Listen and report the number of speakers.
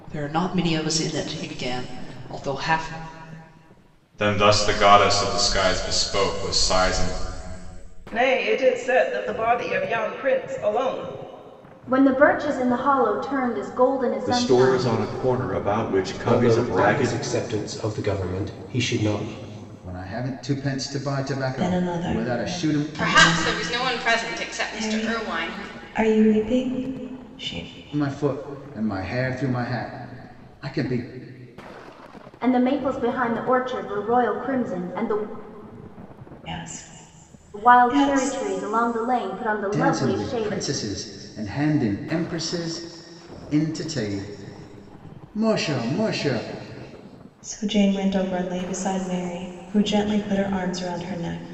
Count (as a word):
nine